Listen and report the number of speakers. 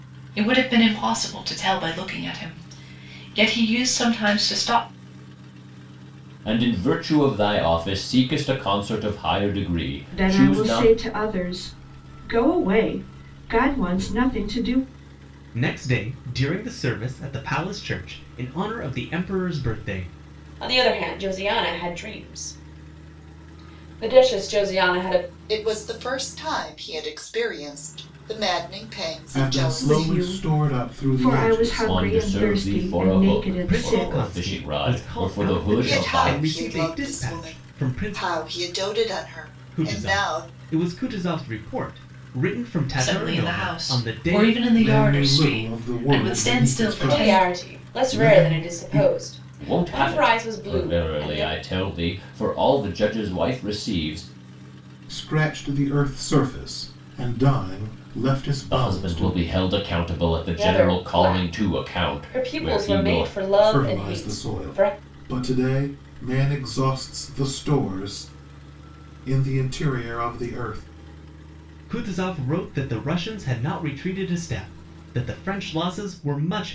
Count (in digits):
7